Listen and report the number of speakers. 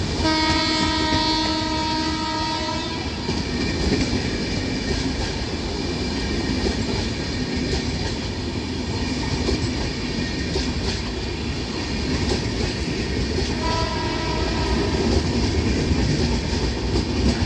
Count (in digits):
0